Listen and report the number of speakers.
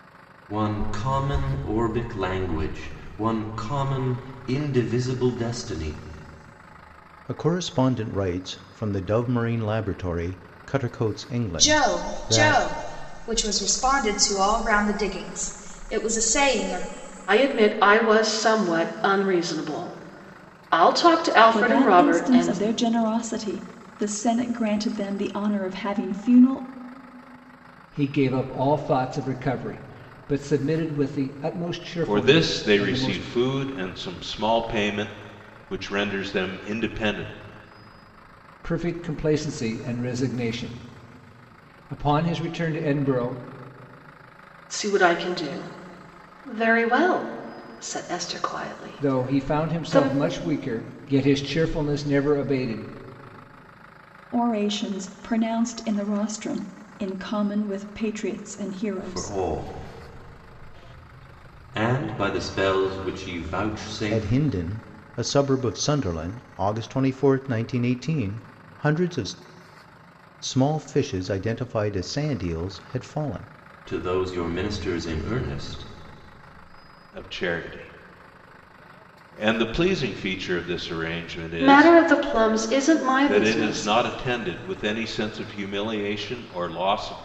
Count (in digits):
7